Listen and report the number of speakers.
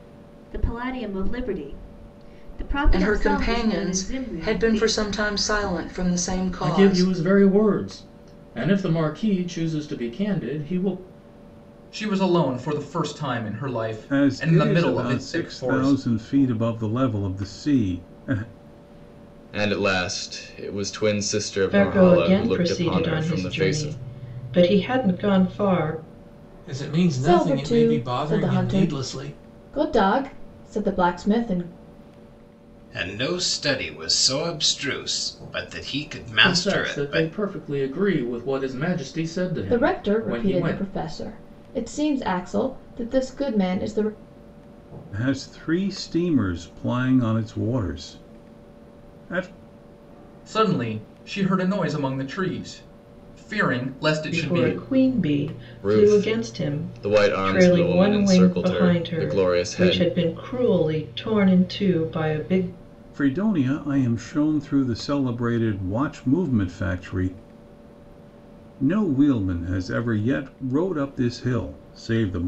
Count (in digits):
10